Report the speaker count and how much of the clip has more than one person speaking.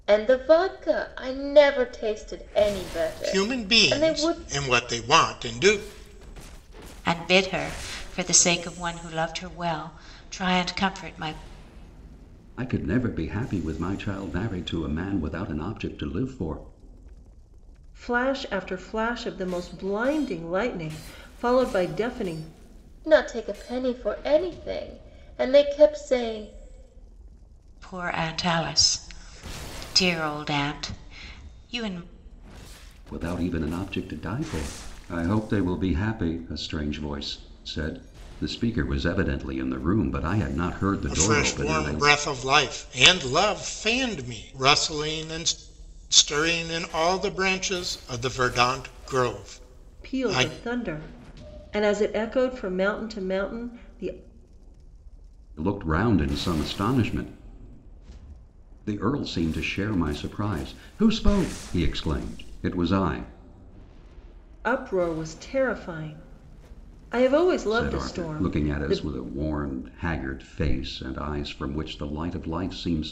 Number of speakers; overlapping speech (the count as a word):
five, about 6%